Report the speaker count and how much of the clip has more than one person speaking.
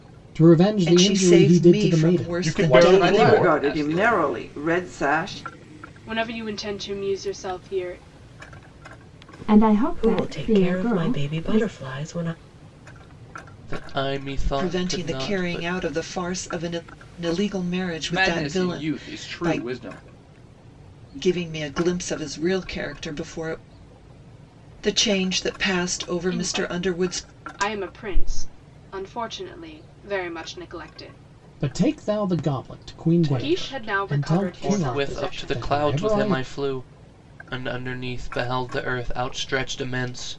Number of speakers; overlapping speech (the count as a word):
nine, about 31%